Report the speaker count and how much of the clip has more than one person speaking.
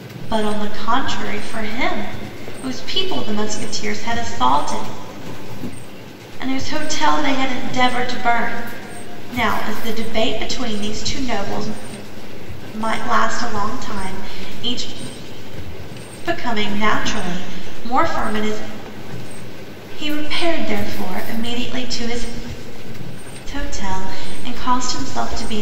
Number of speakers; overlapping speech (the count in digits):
1, no overlap